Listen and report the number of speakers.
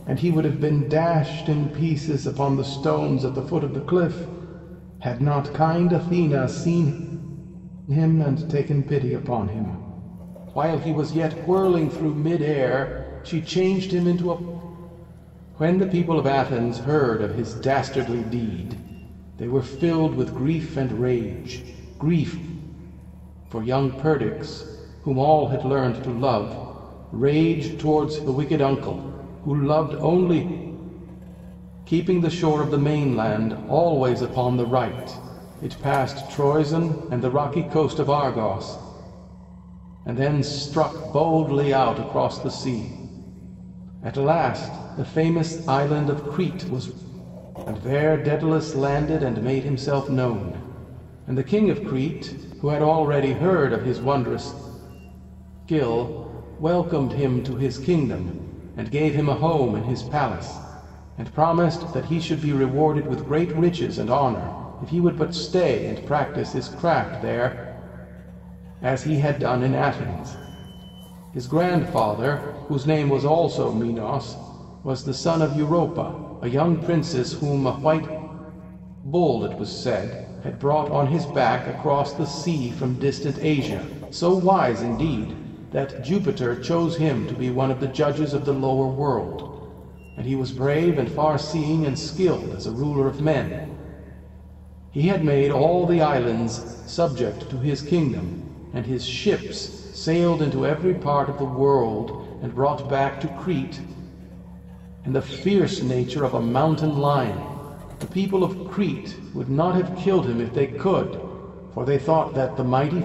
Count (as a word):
one